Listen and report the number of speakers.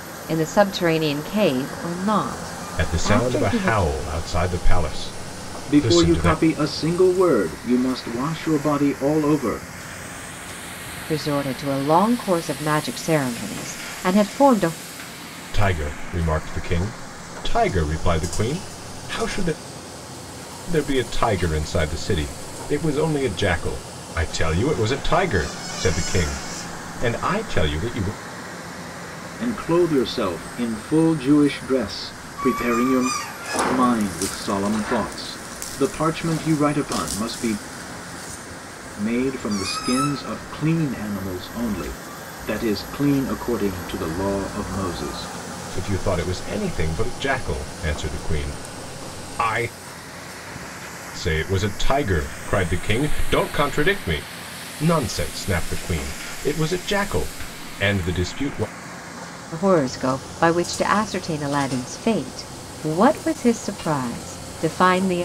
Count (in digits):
3